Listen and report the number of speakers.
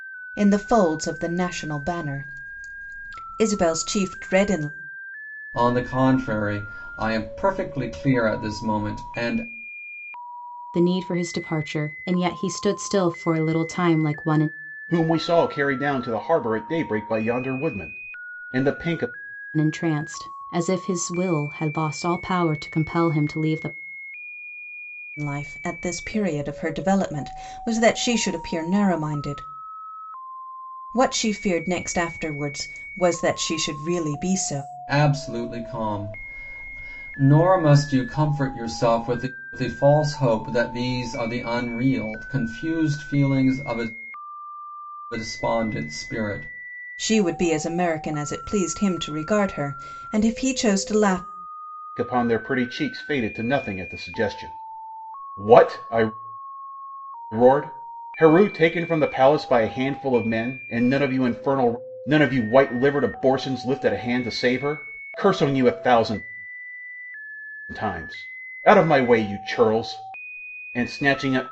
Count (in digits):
4